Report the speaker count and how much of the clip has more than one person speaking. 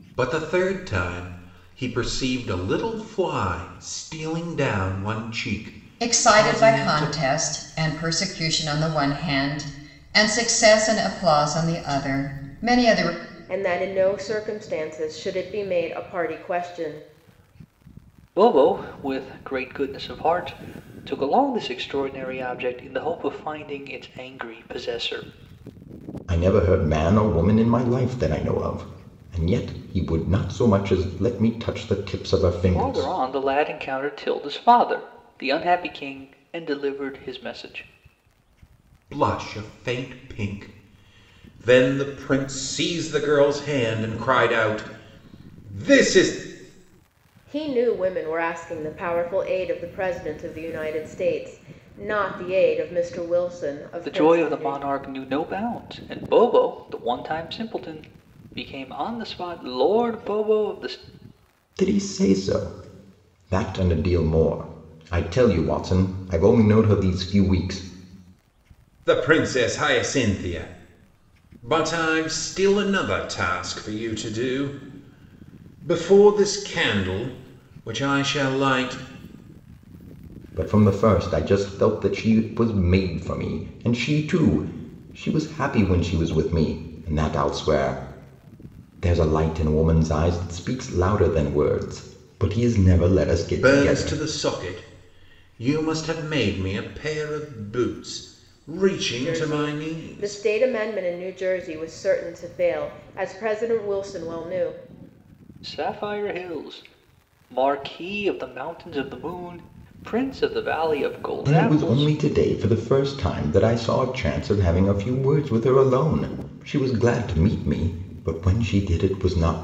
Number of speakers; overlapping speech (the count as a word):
five, about 4%